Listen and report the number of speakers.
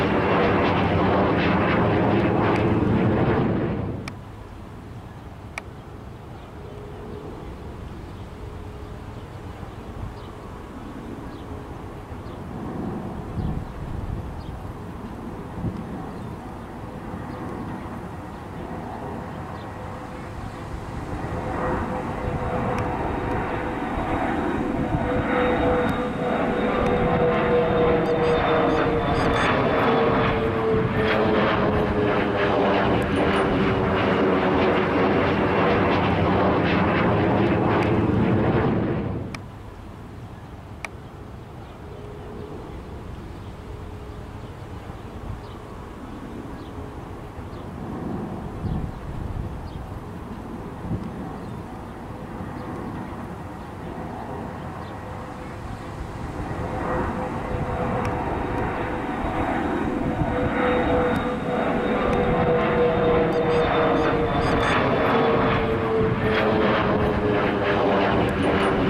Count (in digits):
0